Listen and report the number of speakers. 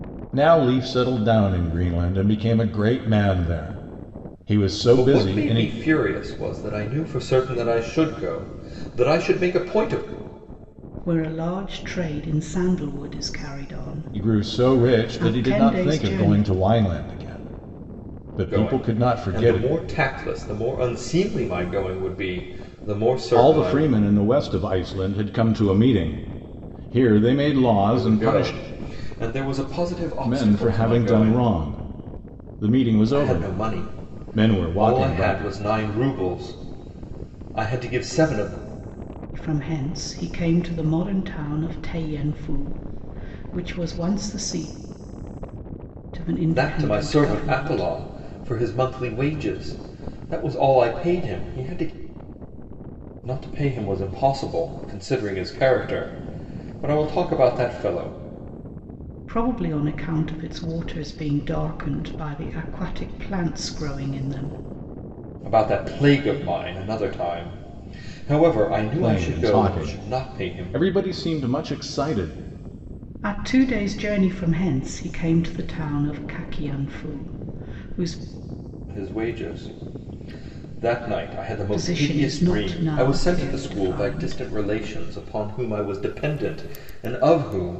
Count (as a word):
three